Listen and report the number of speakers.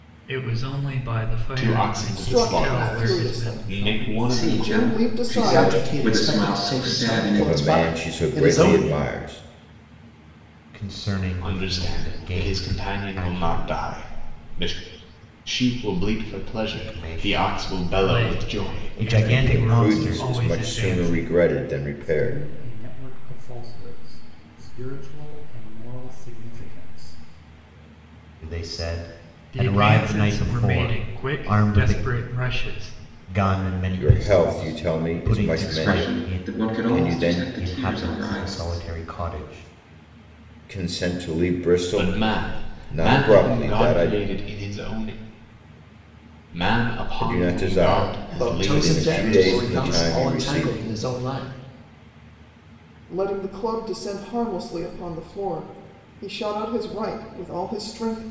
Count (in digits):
8